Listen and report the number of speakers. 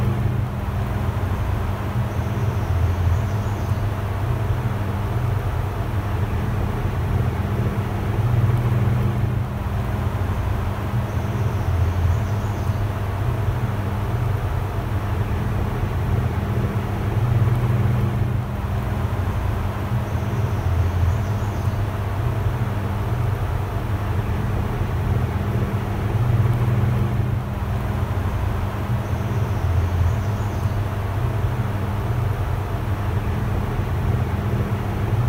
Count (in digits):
0